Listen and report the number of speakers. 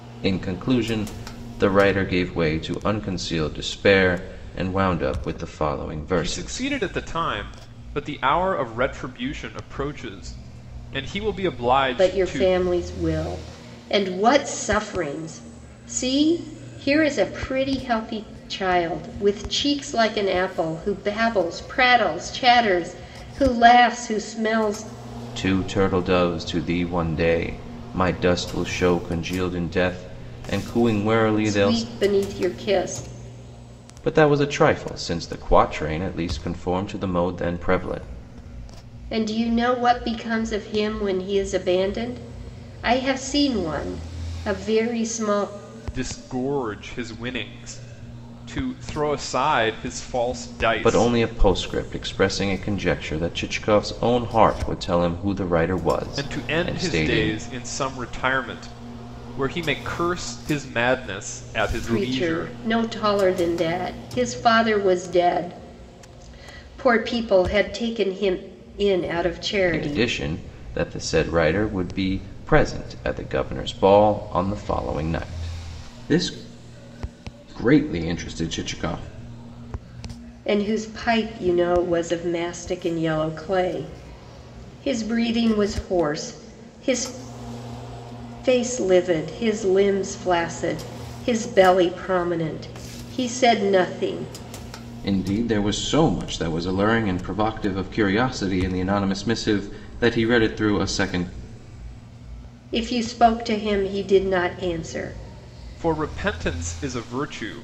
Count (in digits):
3